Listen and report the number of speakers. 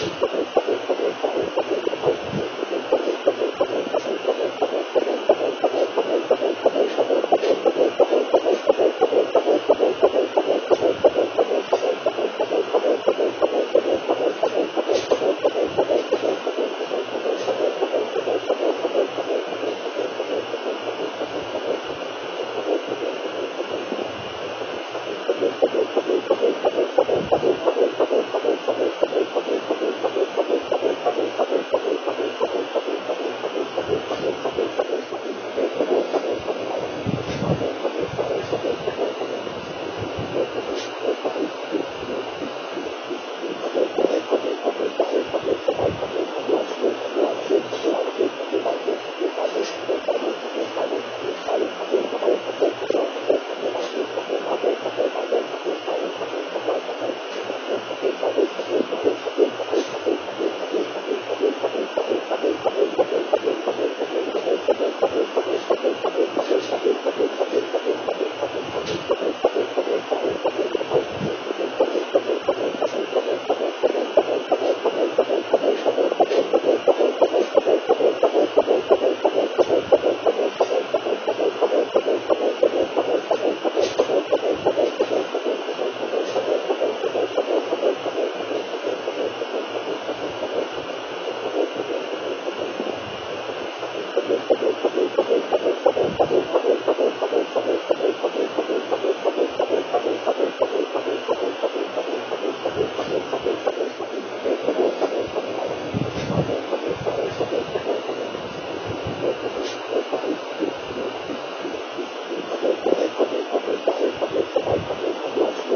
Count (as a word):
zero